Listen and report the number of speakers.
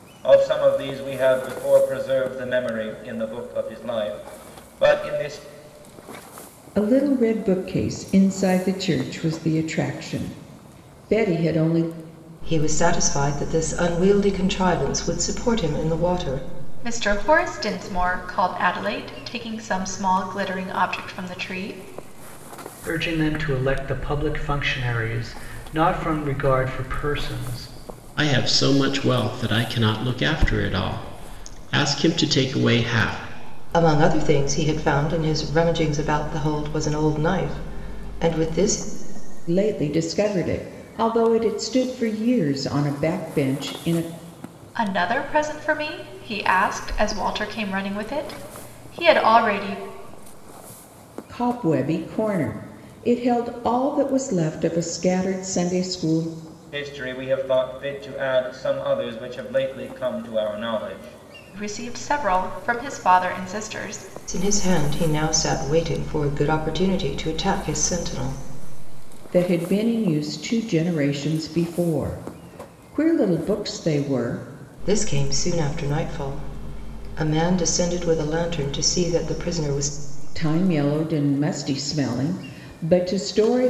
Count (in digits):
6